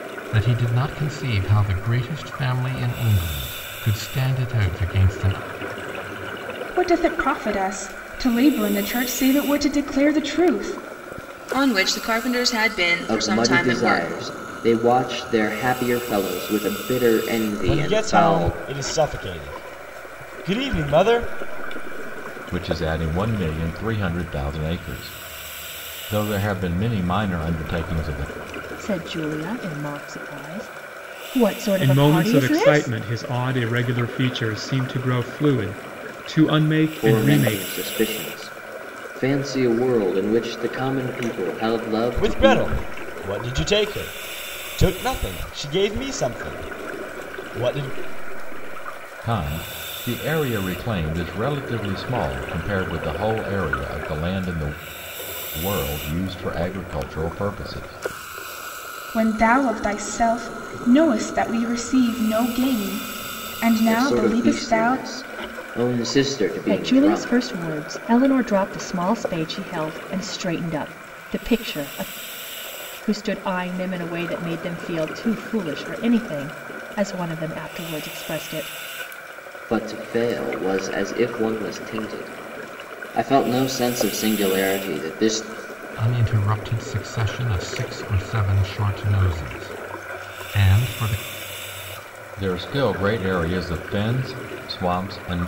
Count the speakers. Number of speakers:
8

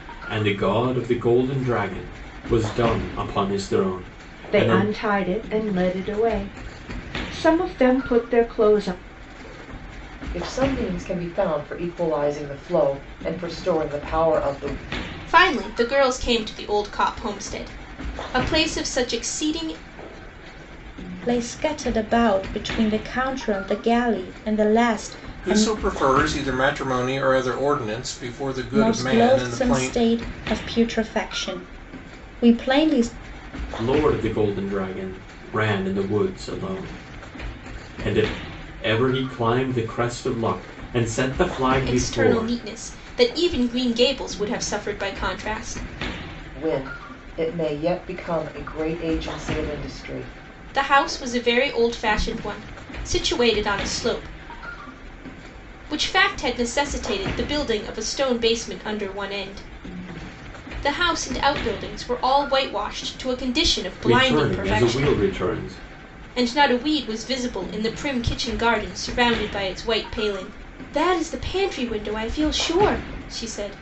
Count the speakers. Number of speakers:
6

